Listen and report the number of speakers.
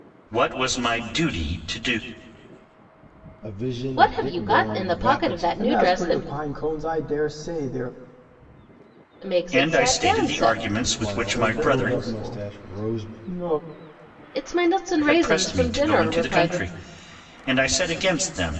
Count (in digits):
4